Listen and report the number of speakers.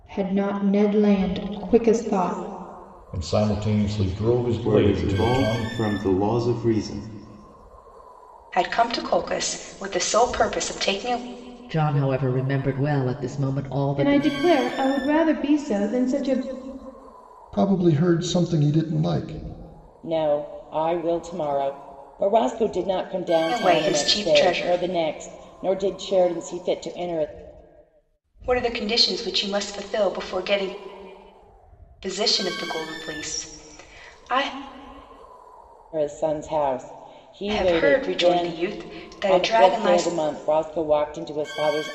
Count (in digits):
8